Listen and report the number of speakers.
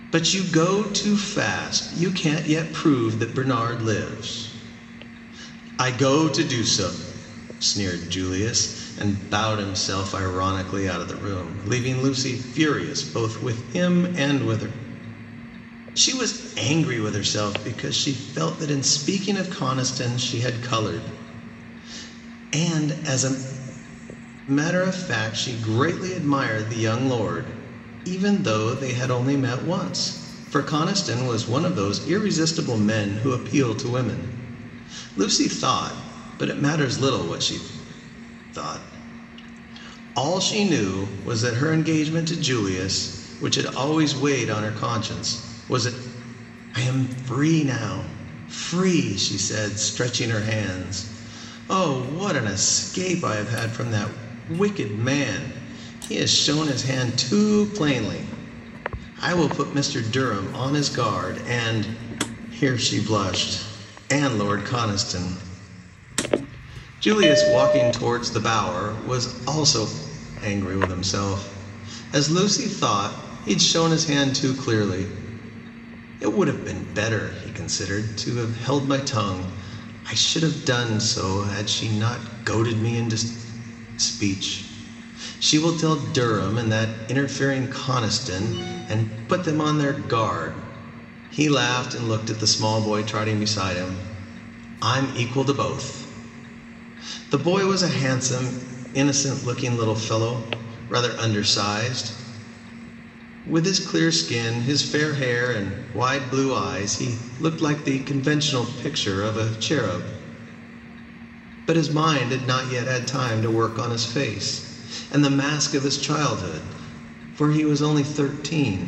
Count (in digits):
1